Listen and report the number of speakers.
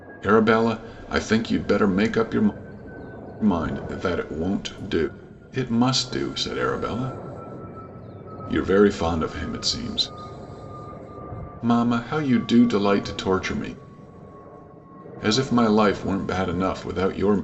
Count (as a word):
one